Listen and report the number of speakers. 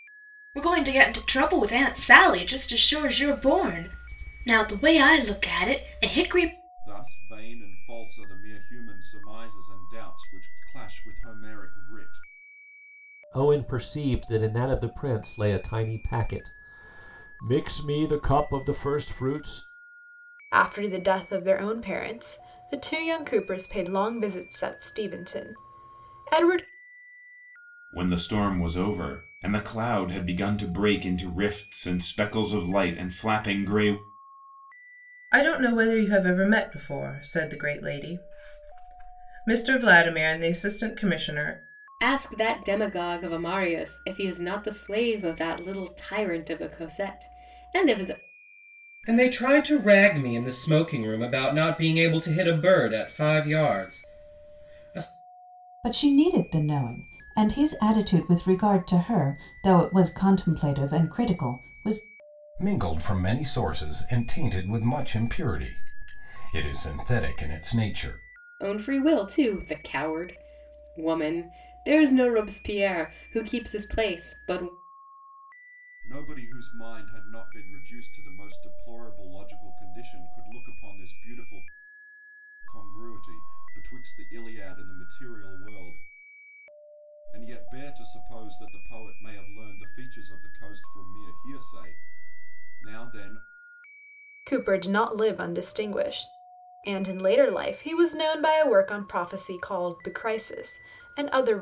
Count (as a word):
ten